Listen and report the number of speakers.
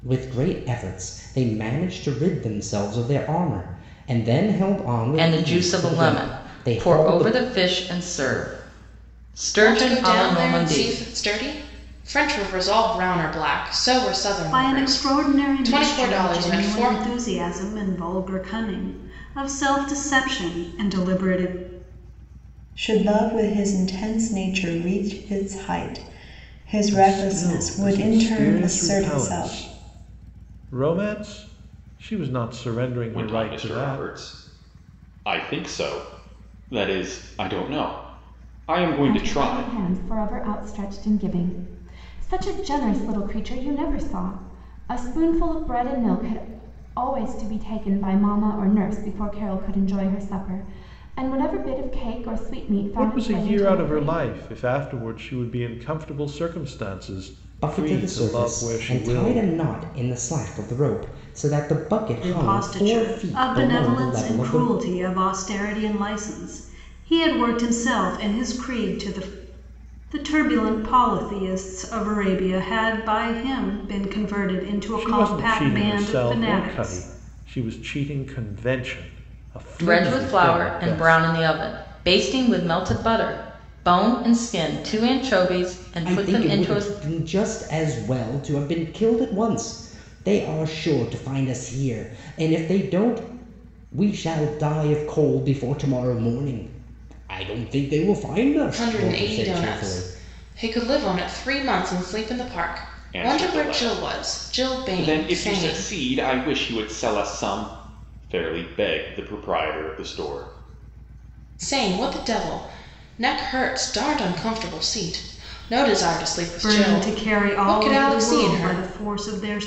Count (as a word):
eight